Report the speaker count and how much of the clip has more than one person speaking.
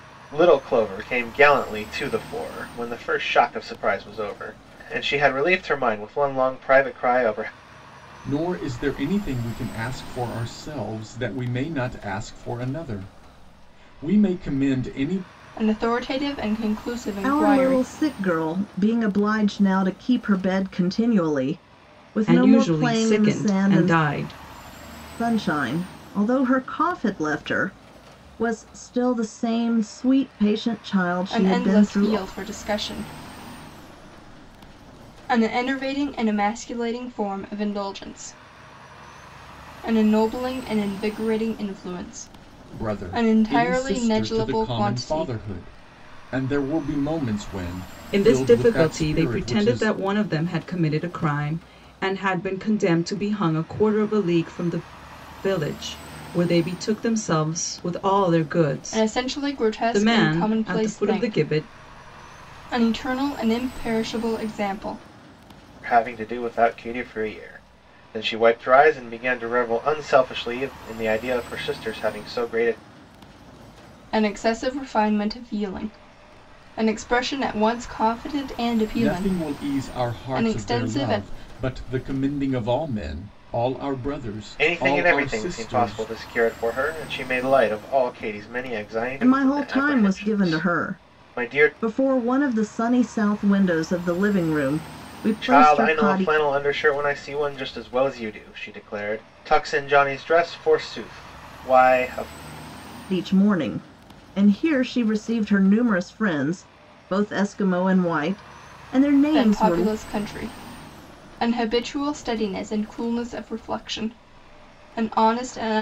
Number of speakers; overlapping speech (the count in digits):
5, about 16%